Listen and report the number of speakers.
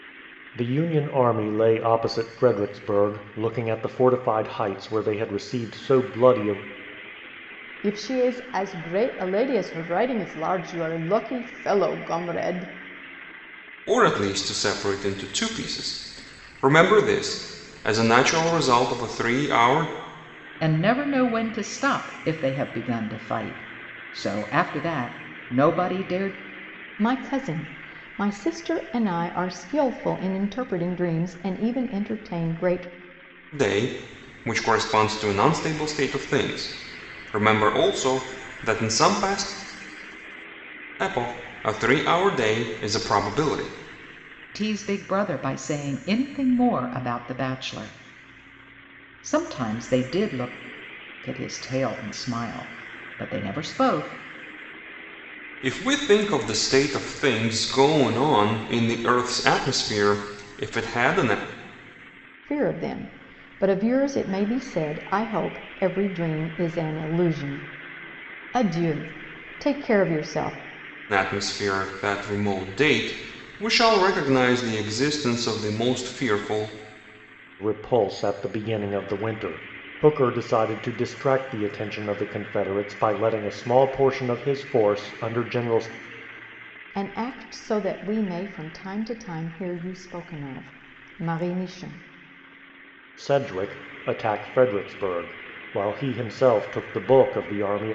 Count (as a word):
four